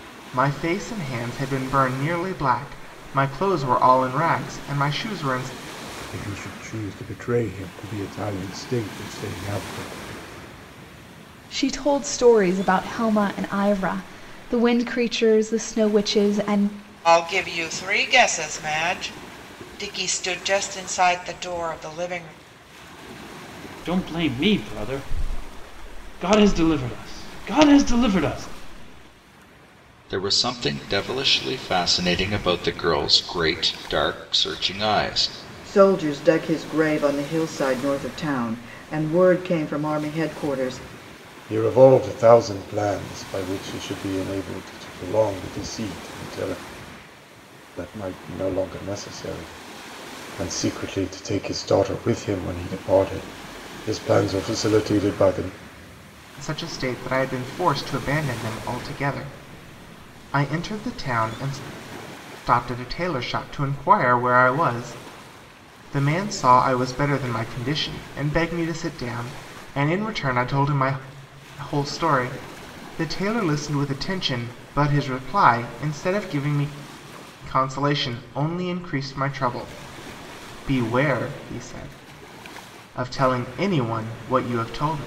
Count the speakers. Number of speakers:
7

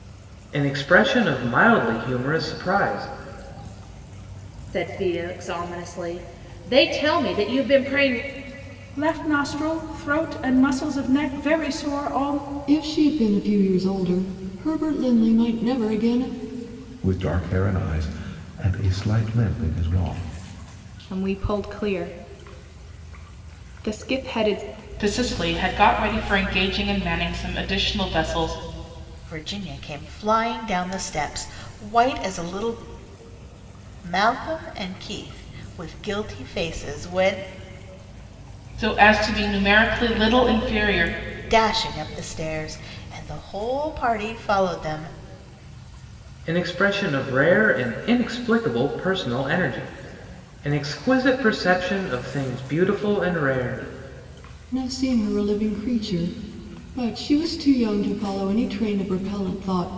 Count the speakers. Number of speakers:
8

